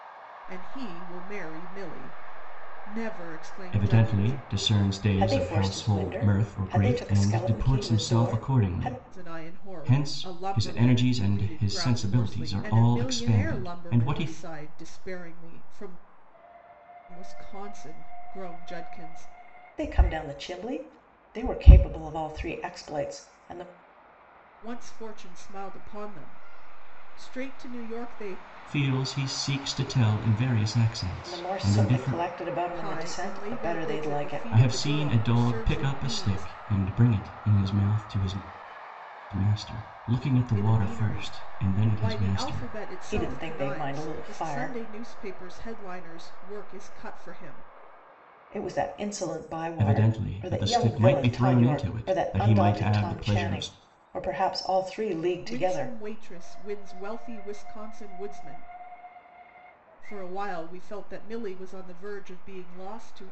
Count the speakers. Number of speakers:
three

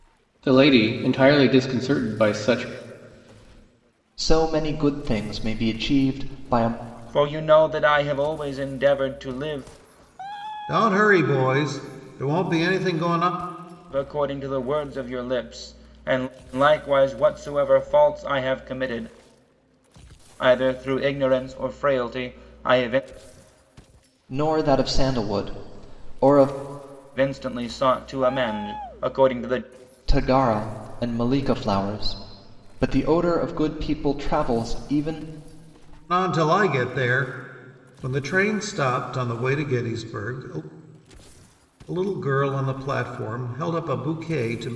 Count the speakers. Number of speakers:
four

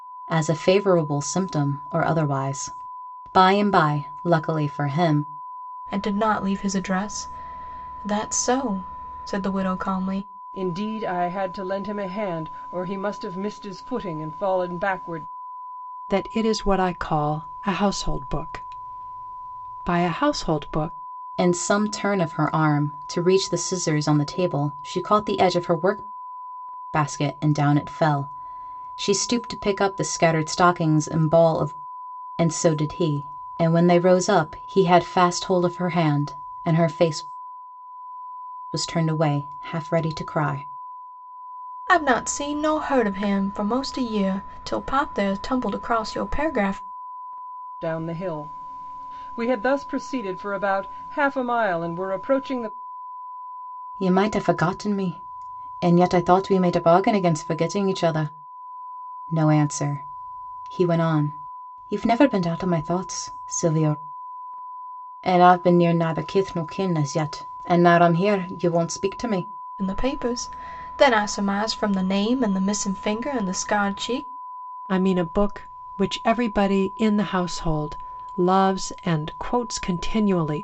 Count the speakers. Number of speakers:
four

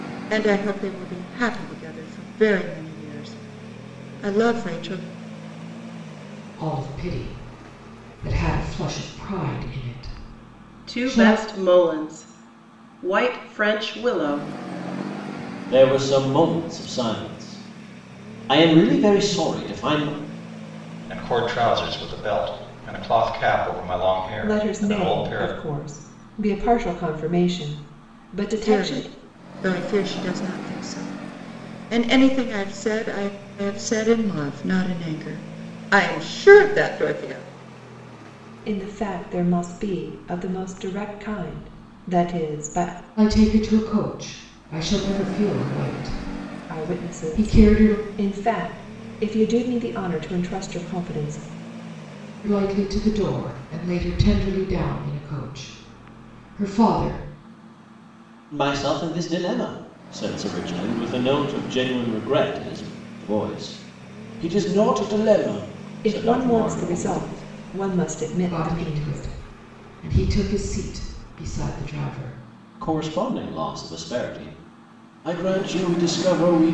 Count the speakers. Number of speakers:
six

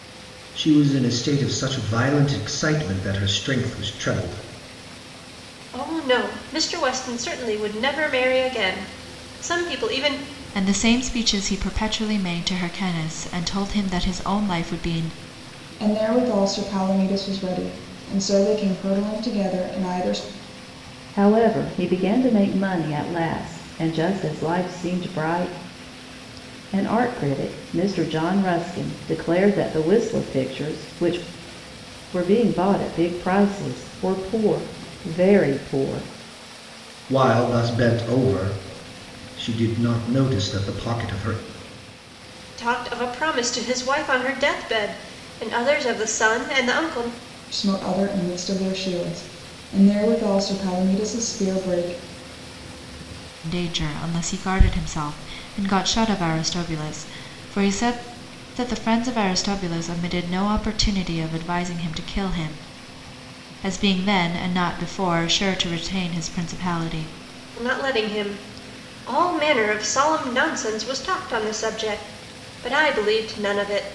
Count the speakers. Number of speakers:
five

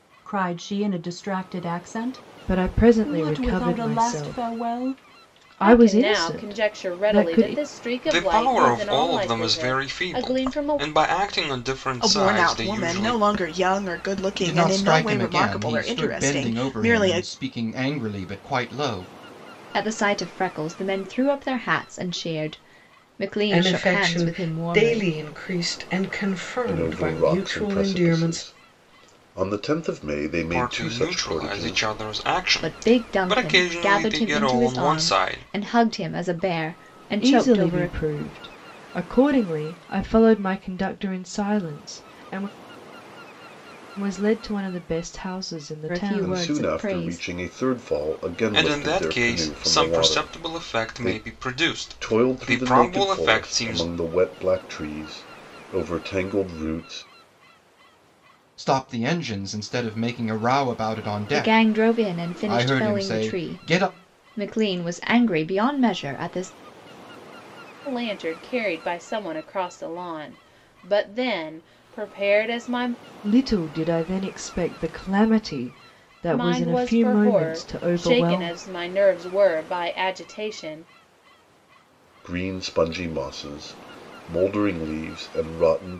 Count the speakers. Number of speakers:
nine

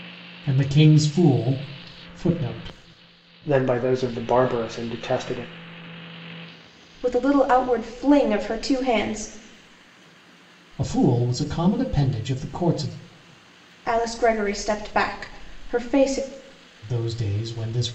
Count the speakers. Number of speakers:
three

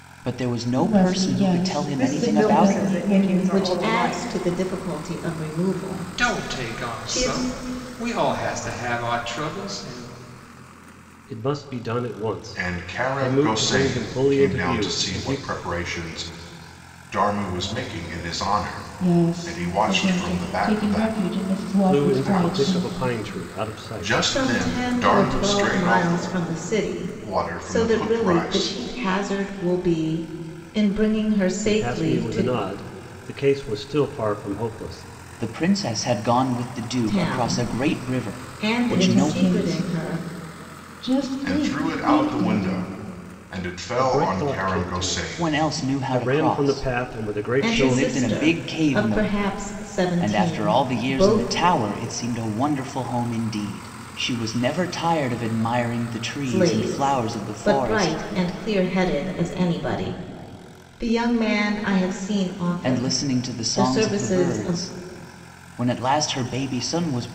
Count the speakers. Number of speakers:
seven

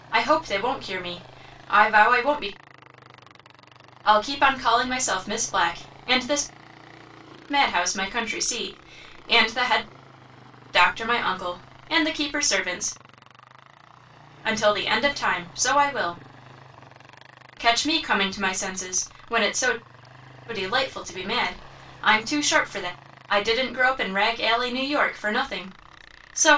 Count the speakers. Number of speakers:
one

